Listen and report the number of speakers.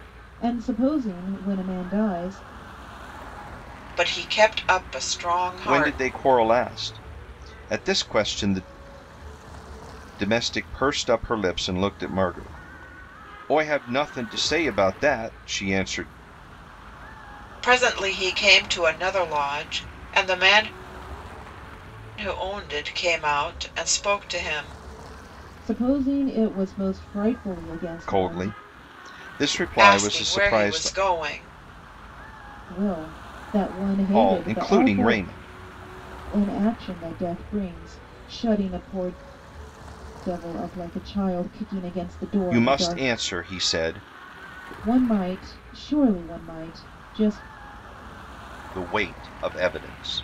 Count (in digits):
3